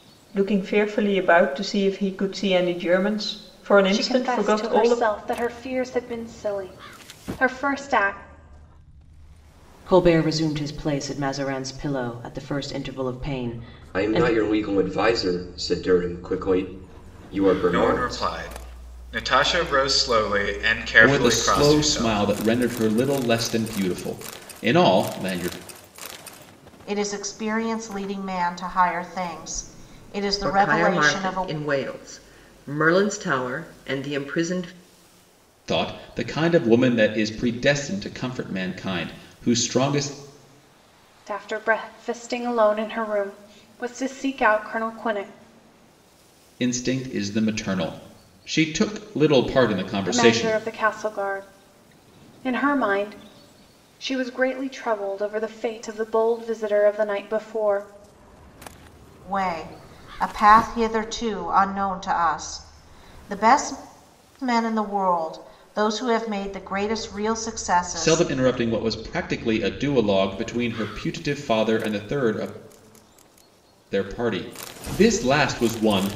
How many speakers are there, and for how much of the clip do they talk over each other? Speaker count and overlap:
eight, about 7%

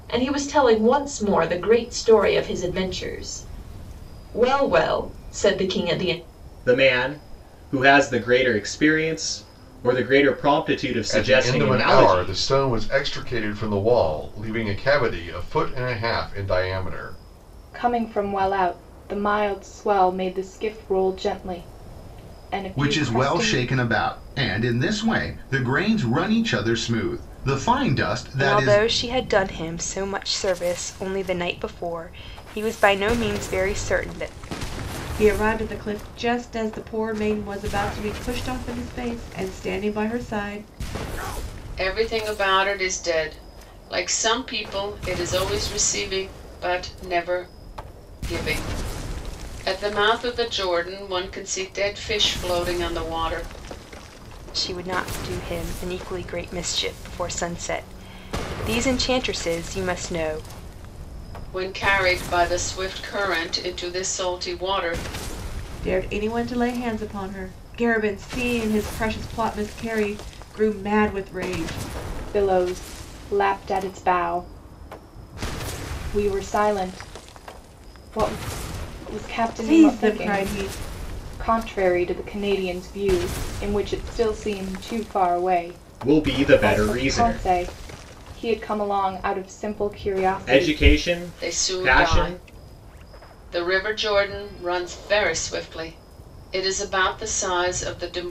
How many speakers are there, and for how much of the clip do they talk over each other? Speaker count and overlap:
eight, about 7%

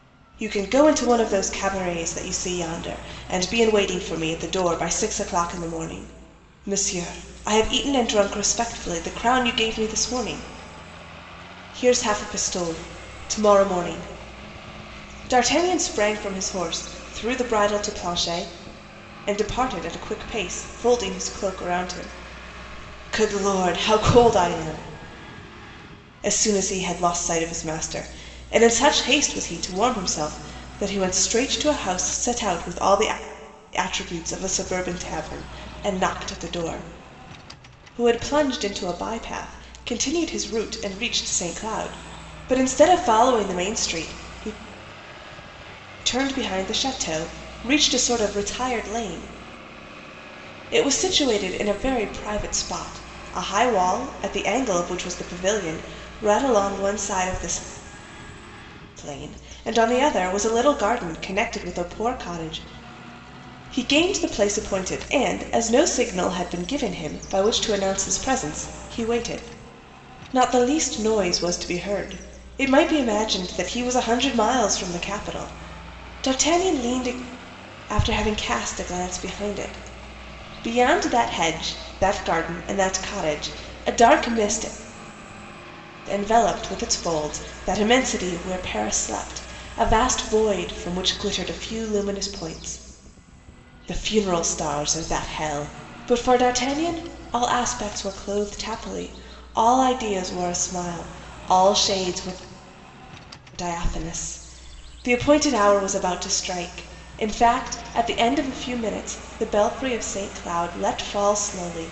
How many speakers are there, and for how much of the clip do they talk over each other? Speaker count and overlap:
one, no overlap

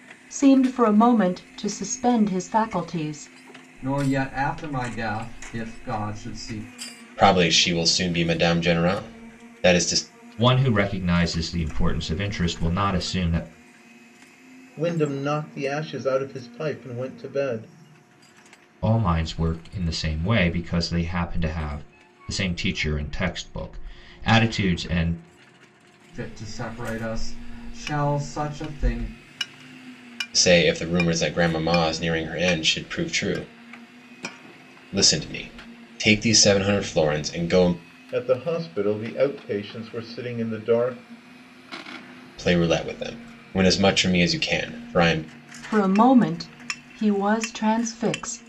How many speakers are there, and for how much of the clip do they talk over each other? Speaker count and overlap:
five, no overlap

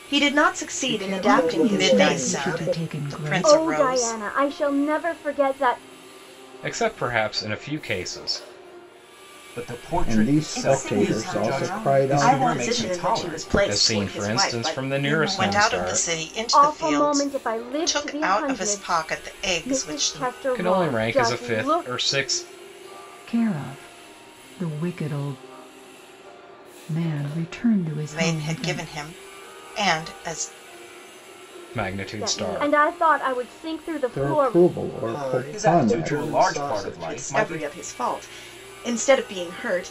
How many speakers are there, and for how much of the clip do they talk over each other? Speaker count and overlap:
nine, about 45%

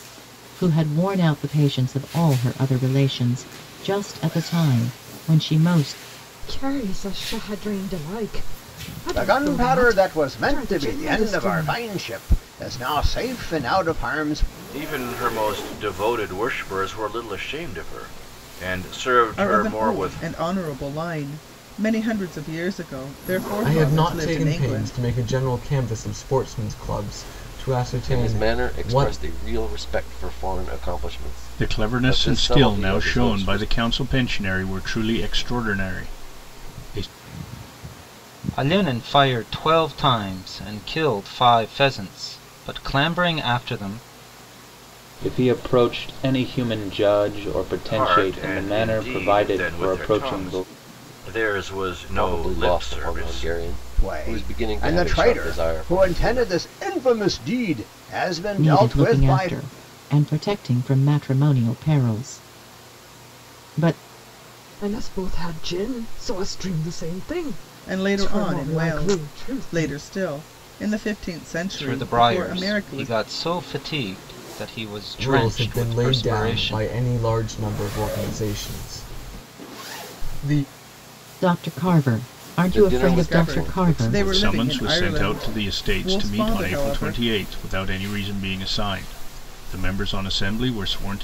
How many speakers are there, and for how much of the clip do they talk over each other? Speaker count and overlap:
ten, about 29%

